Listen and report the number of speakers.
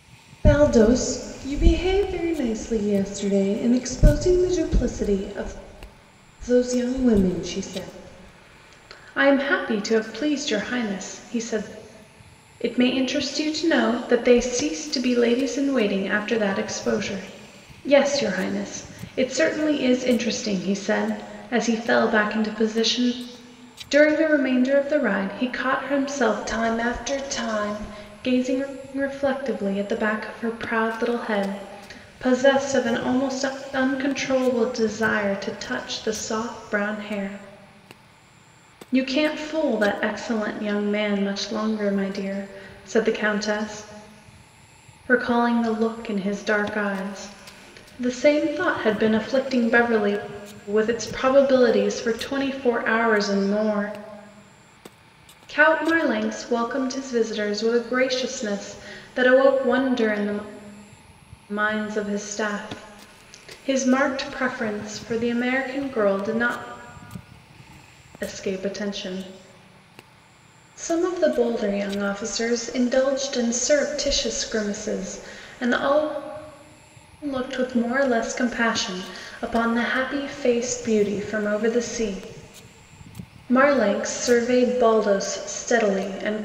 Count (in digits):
1